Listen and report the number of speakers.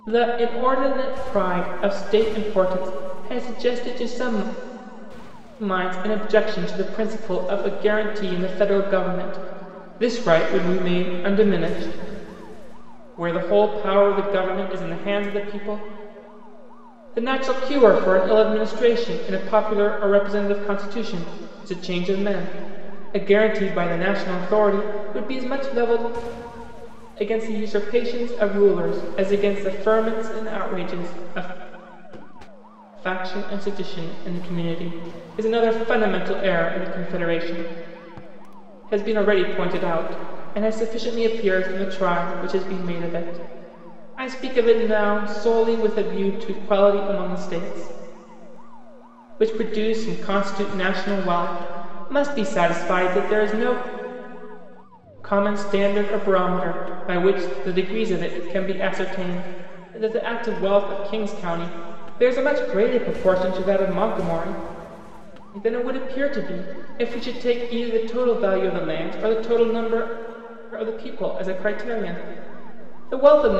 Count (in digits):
1